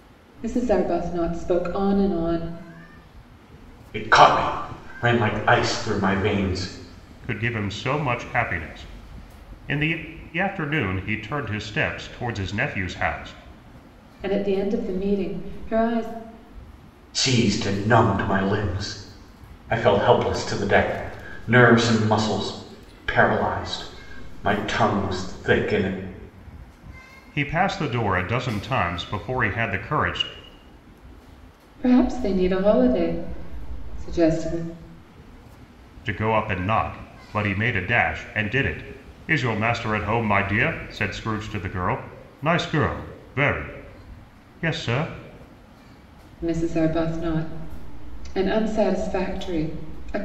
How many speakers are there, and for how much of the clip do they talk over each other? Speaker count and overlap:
three, no overlap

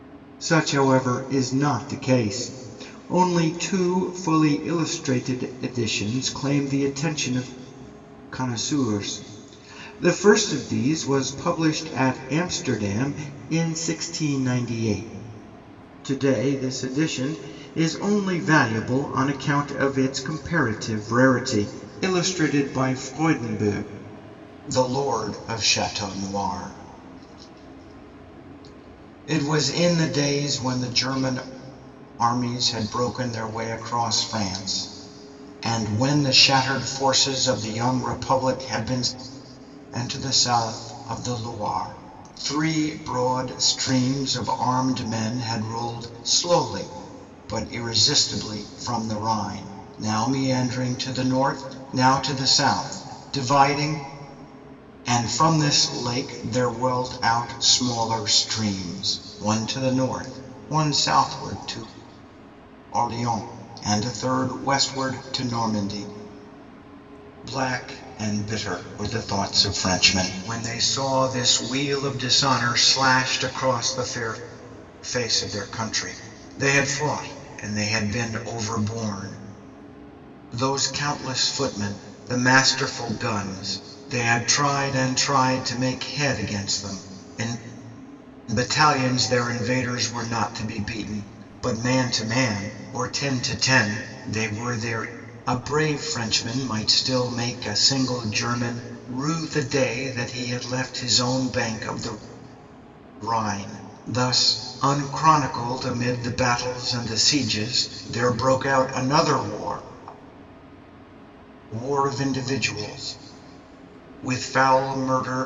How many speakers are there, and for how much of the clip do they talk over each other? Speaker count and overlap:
one, no overlap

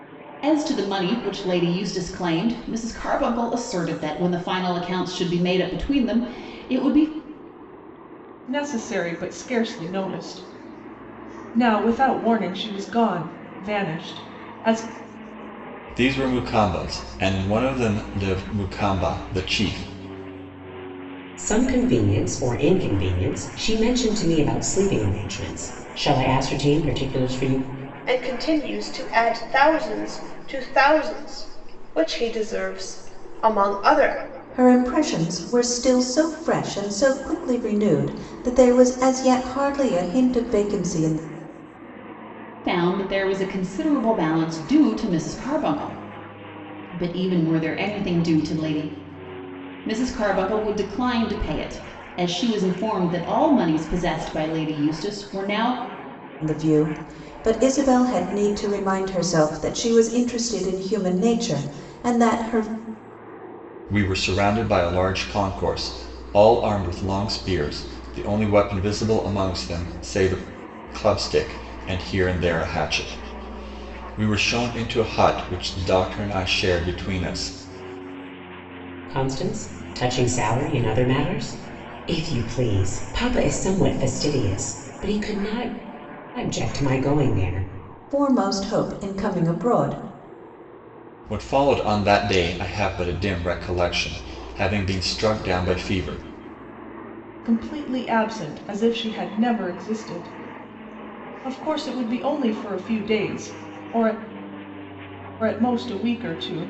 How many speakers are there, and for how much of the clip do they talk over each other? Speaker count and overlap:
six, no overlap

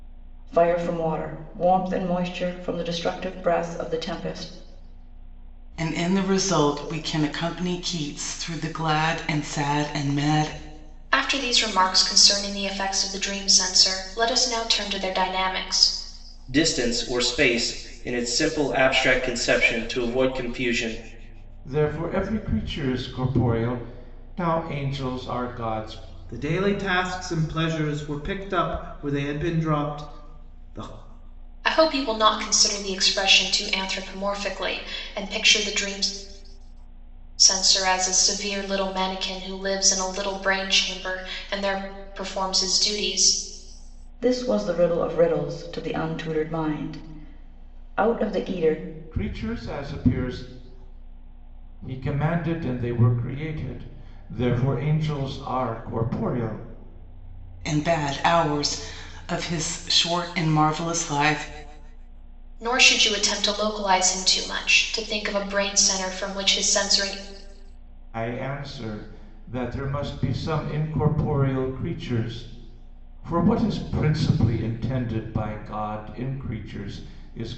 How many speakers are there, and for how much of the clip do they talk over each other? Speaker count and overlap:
six, no overlap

